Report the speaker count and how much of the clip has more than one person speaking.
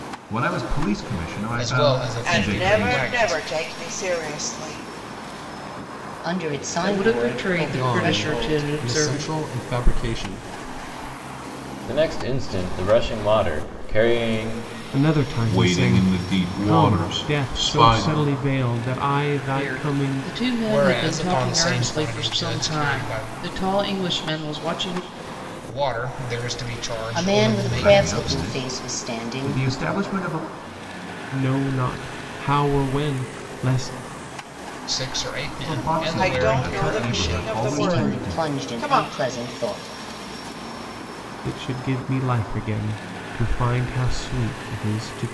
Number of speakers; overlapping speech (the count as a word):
nine, about 36%